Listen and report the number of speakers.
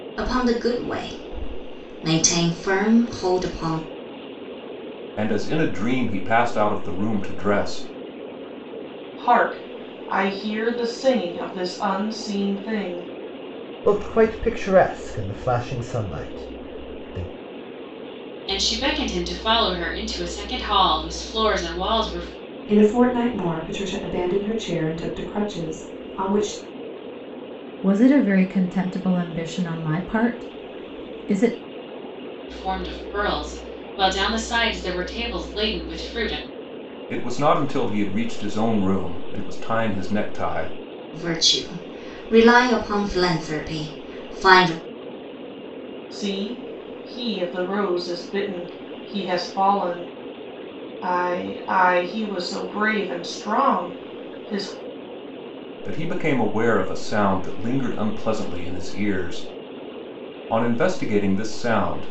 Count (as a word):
seven